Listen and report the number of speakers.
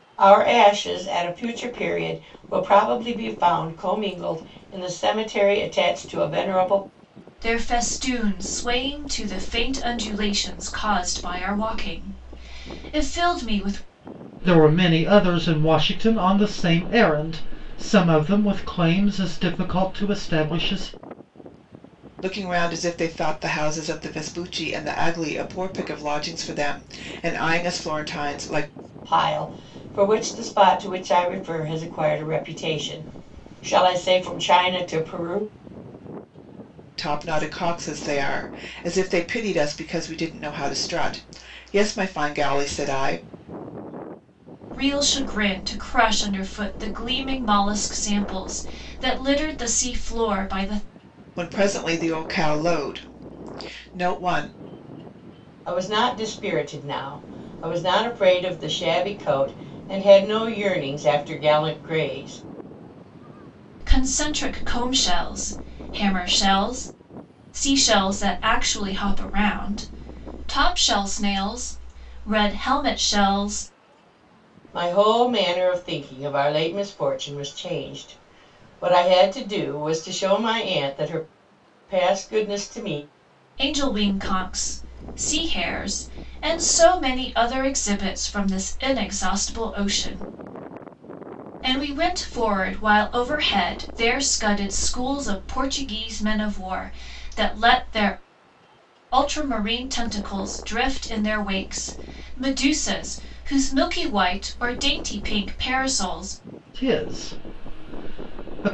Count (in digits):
4